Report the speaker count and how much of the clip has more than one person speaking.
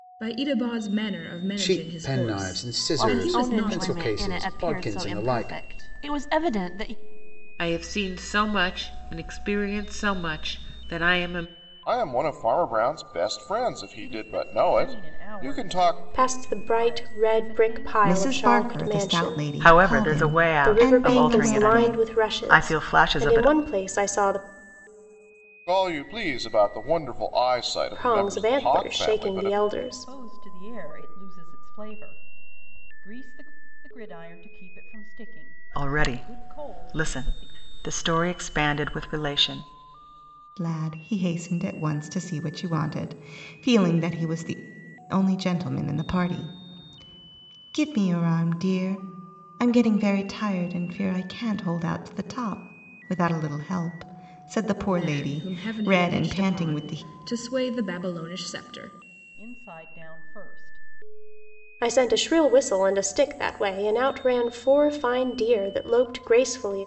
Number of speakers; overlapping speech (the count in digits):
9, about 30%